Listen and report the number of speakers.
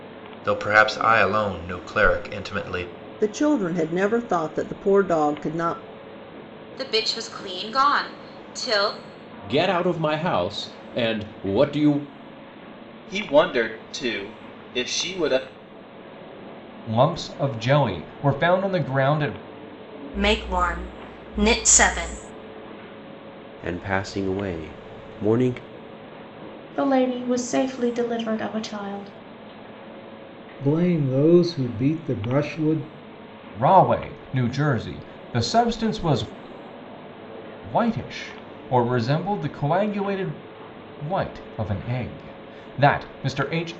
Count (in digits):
10